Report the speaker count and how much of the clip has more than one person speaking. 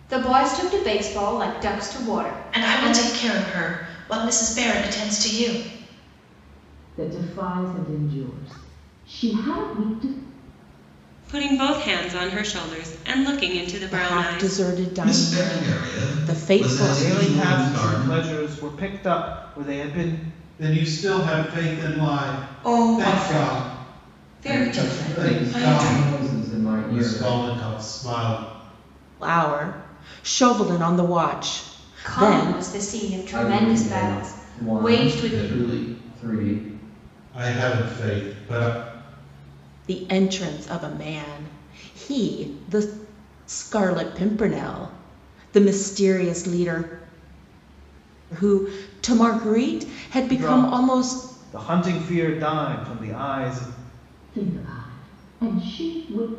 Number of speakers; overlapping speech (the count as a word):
ten, about 24%